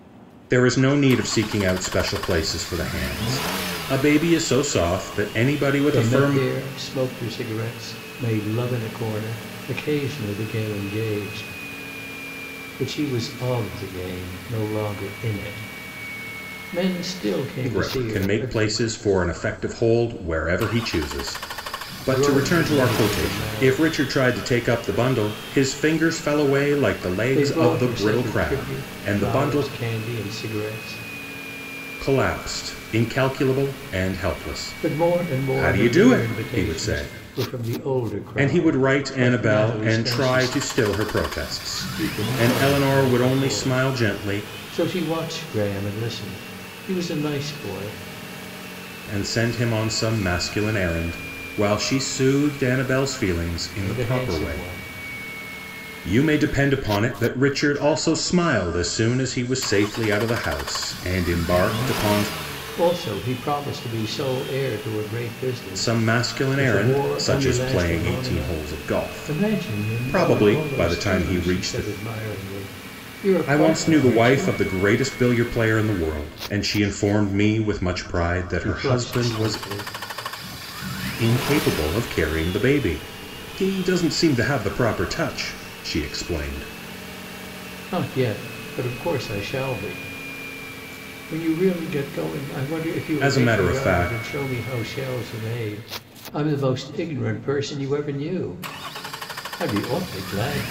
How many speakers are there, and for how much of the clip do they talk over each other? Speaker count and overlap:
two, about 23%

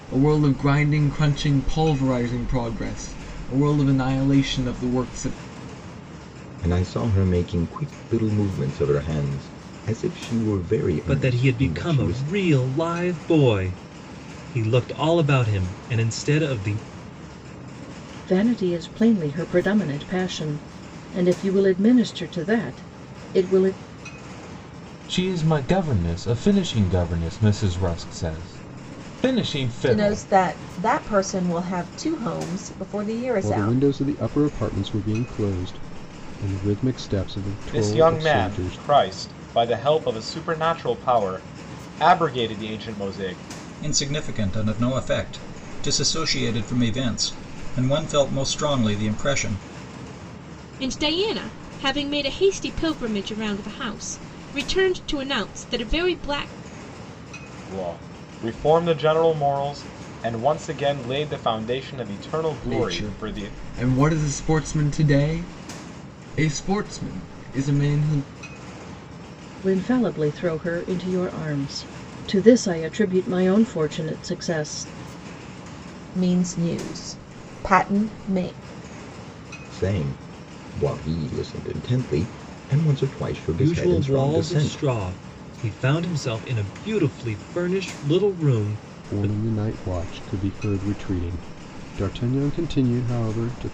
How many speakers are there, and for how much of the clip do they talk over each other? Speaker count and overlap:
ten, about 6%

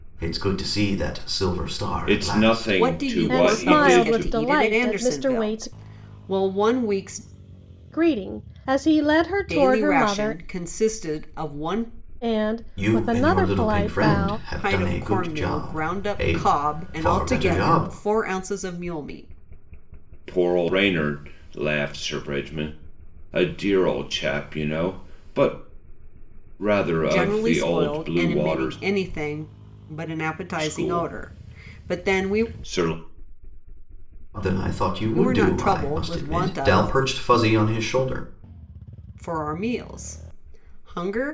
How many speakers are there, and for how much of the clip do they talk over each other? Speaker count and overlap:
four, about 37%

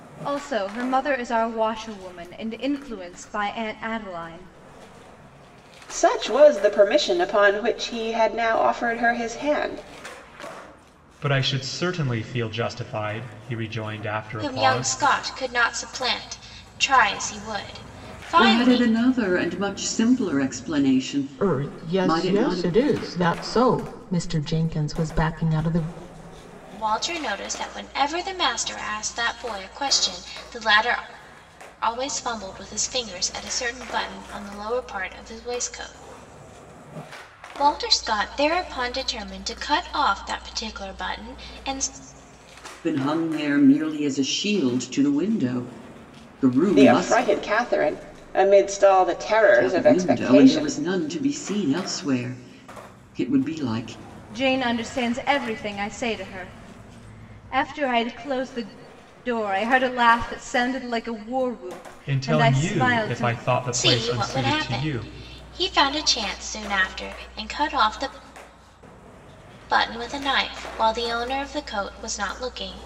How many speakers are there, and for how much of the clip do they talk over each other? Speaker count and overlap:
six, about 10%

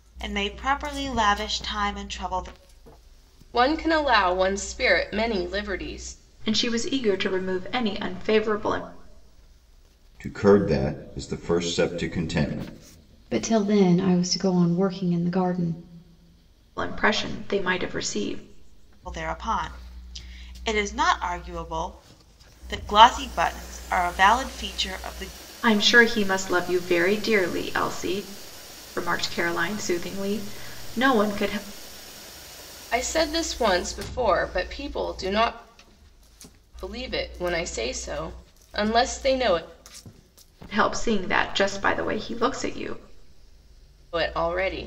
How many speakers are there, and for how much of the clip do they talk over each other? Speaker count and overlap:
five, no overlap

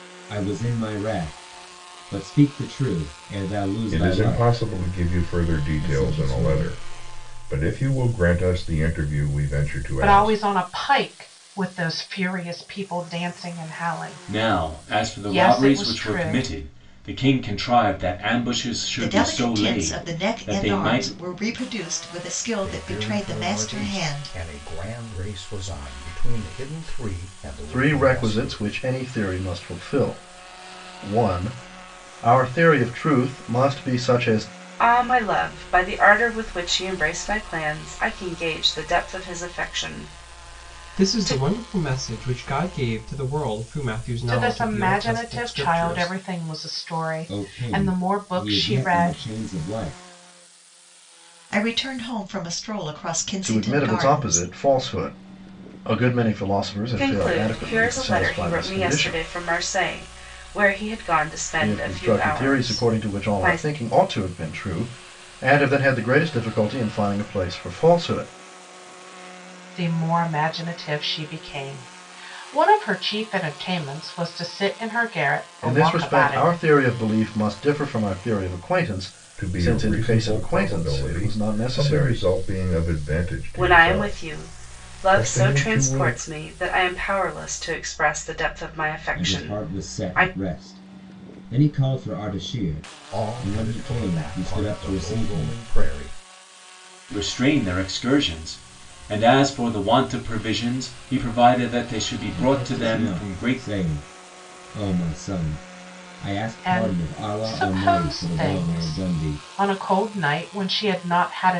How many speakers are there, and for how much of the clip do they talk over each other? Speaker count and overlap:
nine, about 32%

